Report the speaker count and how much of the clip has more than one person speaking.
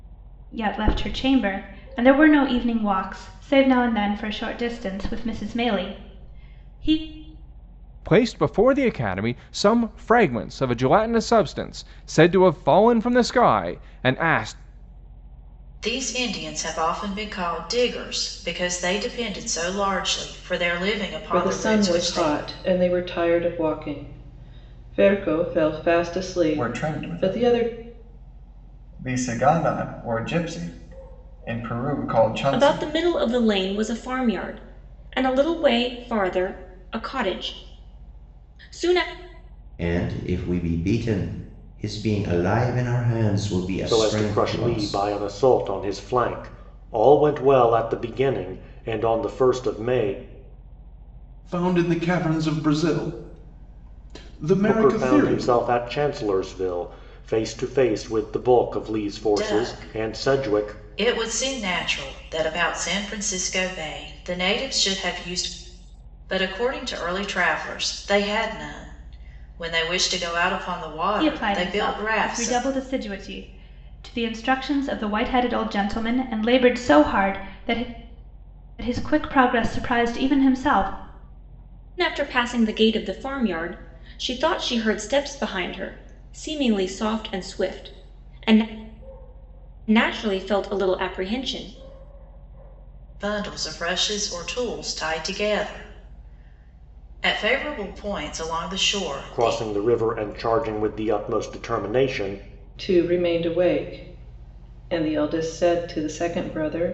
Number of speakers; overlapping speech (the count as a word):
nine, about 8%